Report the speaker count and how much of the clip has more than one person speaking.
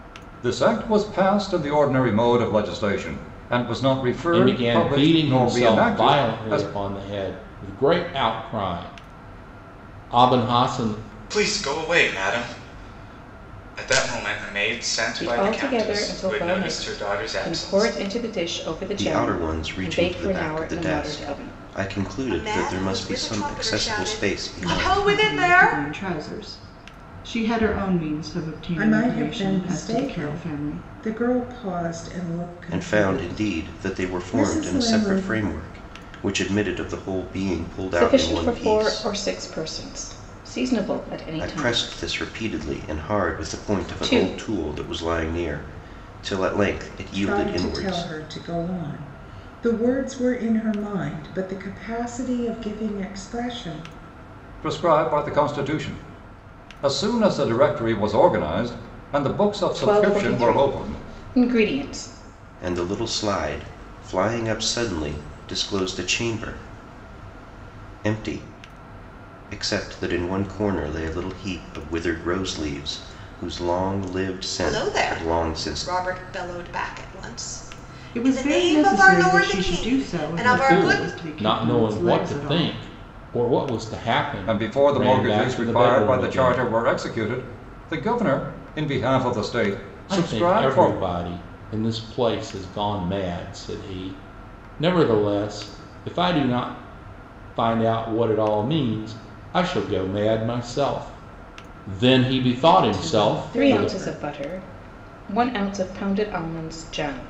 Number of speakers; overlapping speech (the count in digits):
8, about 31%